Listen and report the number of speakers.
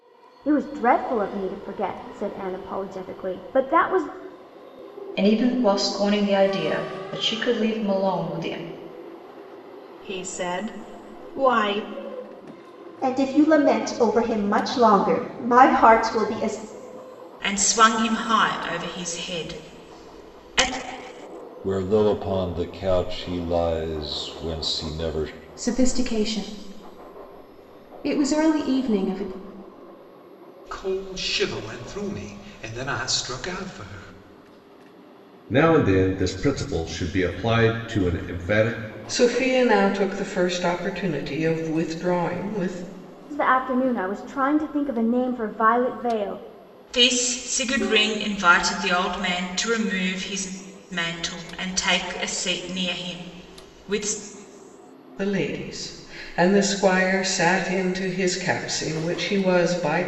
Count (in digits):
10